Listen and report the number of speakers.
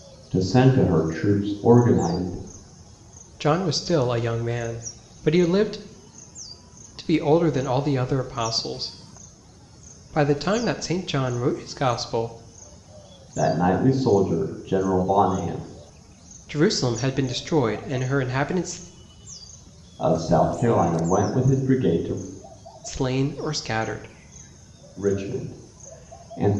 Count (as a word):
two